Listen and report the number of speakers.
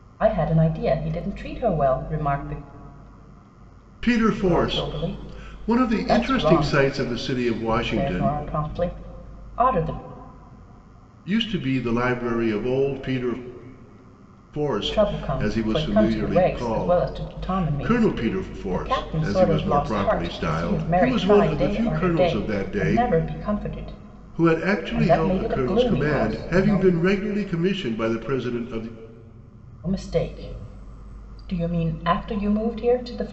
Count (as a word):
two